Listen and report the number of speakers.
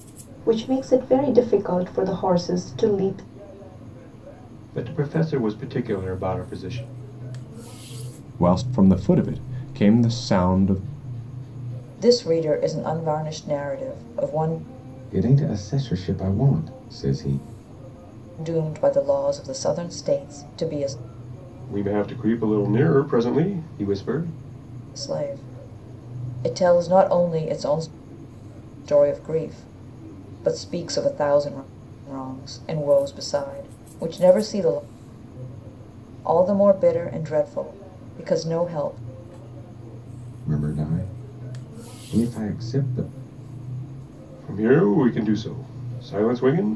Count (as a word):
five